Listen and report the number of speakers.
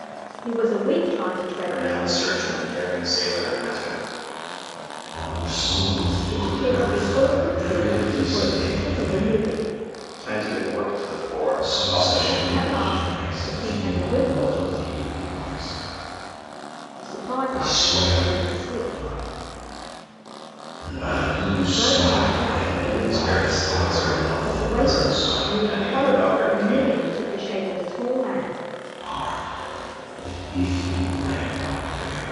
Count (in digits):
3